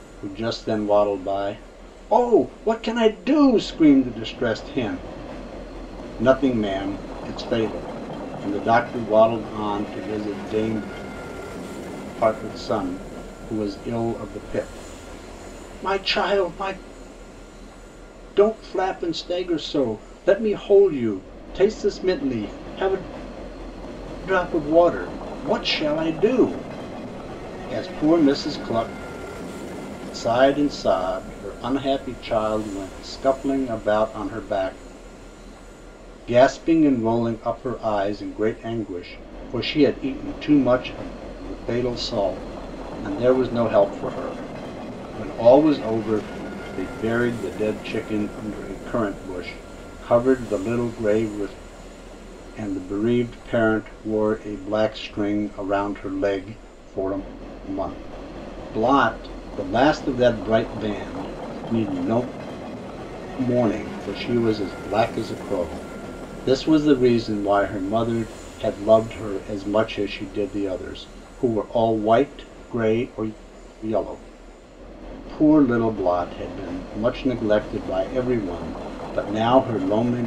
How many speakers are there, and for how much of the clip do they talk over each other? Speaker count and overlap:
1, no overlap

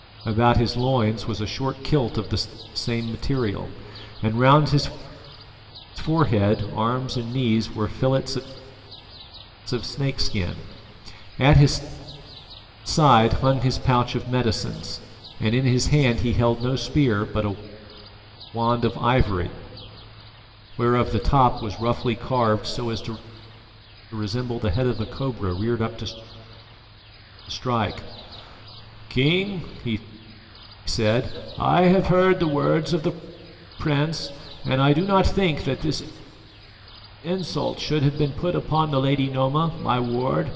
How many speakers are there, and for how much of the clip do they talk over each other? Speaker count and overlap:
1, no overlap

